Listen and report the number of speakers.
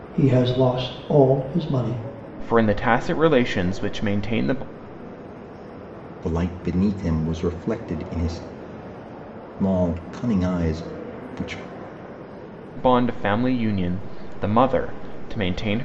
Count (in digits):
3